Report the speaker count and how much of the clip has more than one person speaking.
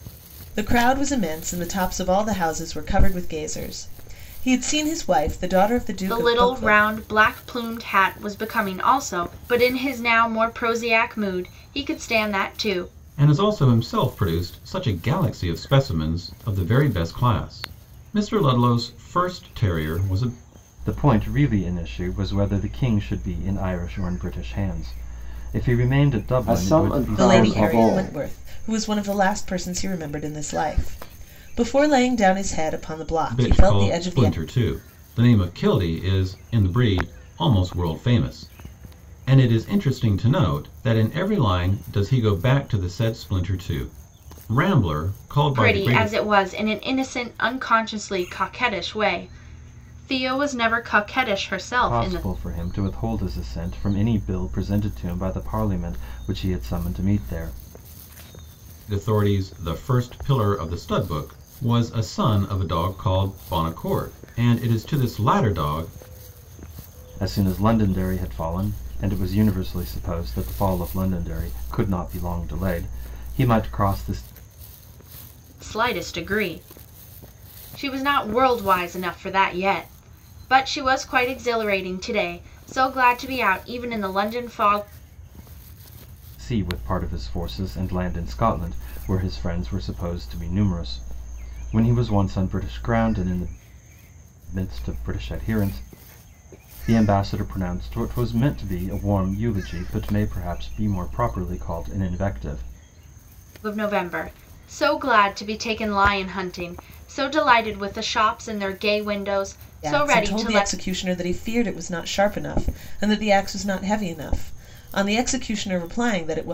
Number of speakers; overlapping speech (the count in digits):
5, about 5%